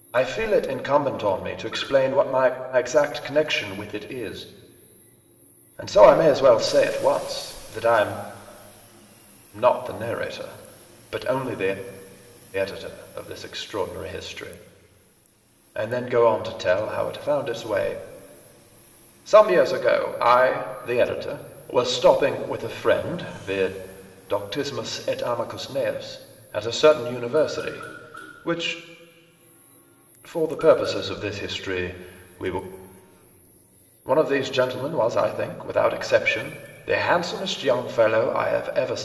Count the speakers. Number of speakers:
one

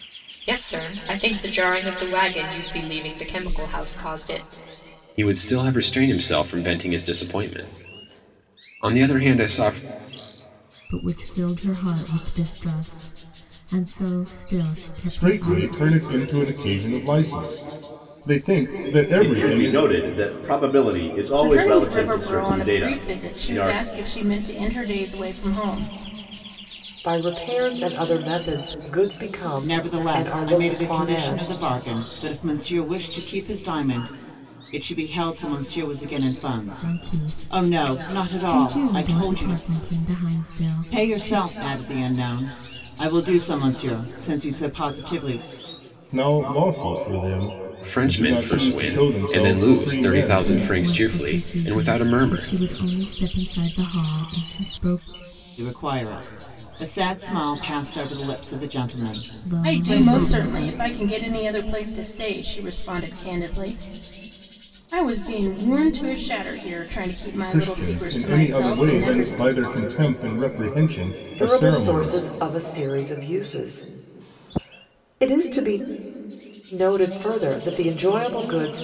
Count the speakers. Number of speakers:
eight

